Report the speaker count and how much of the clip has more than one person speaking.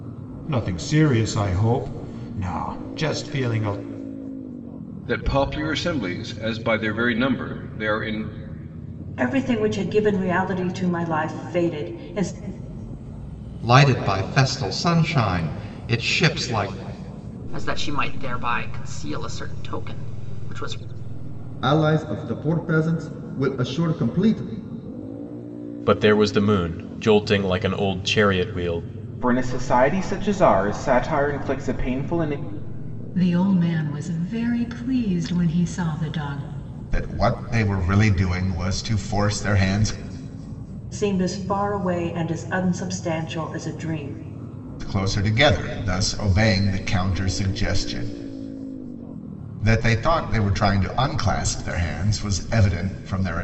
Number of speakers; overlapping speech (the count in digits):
10, no overlap